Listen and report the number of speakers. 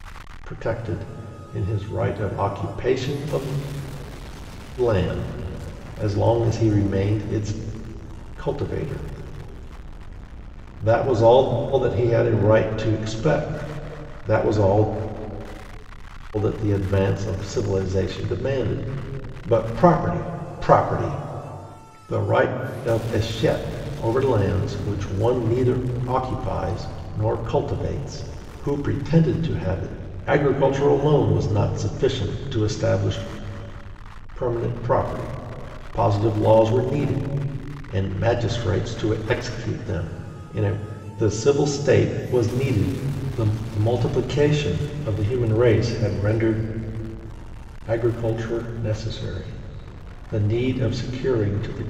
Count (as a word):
one